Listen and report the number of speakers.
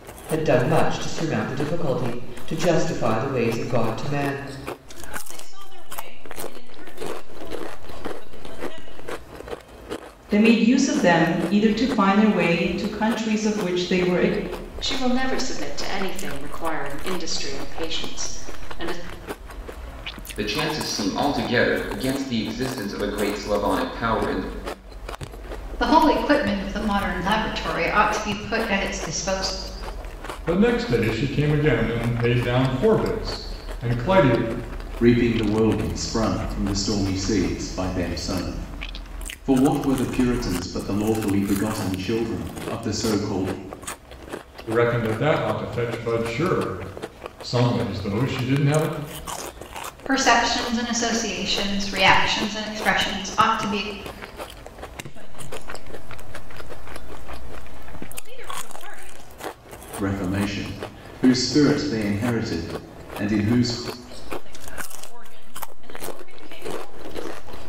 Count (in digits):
8